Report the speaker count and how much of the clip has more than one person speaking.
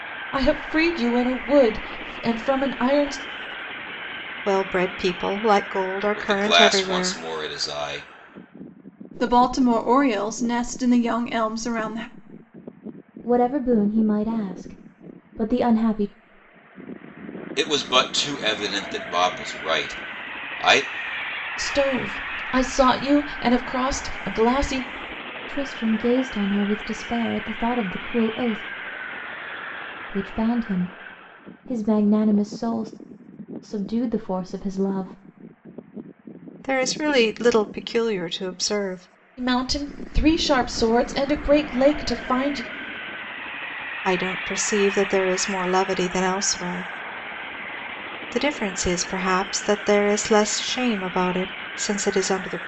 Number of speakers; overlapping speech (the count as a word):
five, about 2%